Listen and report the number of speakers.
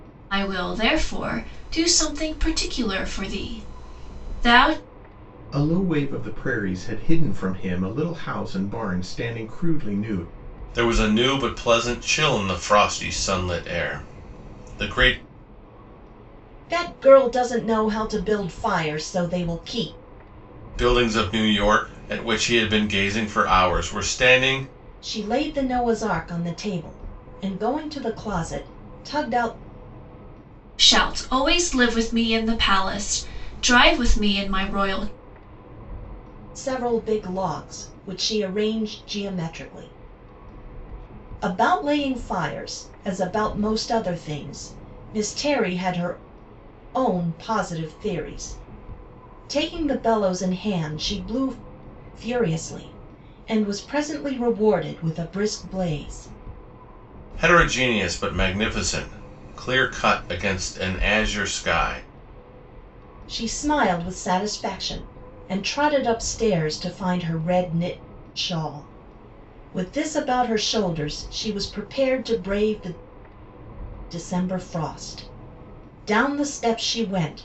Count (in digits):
4